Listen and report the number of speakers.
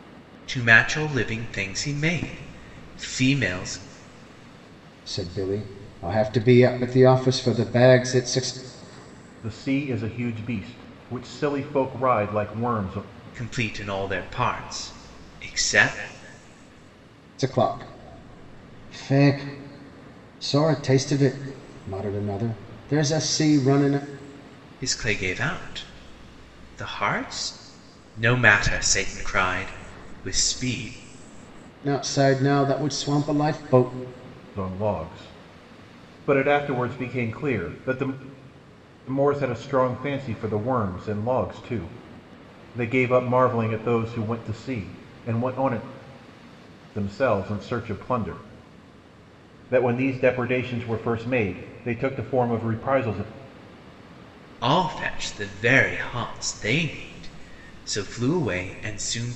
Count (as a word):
three